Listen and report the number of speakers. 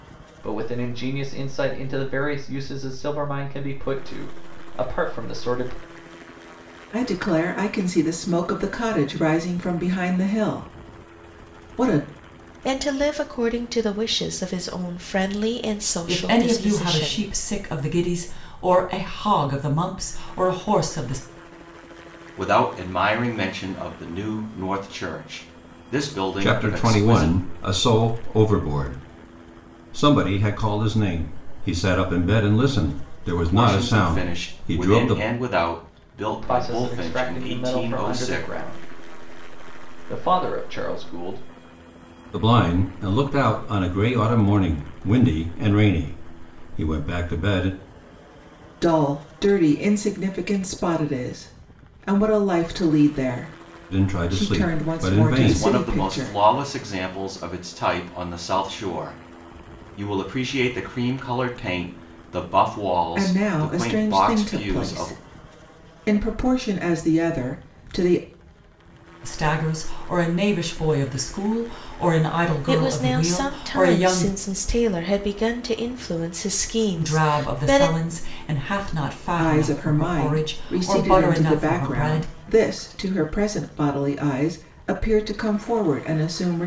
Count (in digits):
6